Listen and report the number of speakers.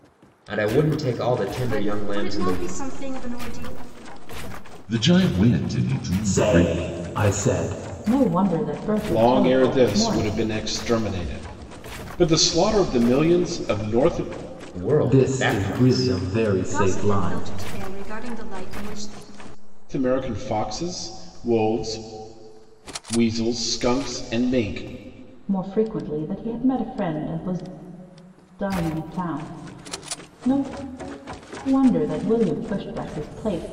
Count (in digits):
6